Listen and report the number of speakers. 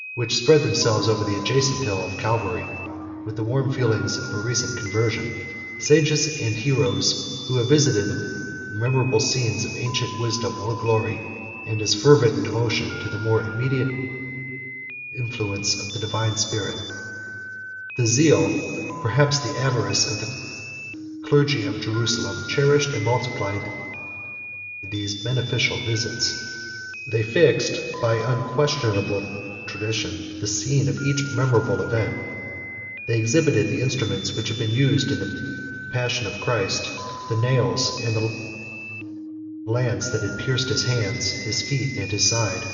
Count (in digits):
1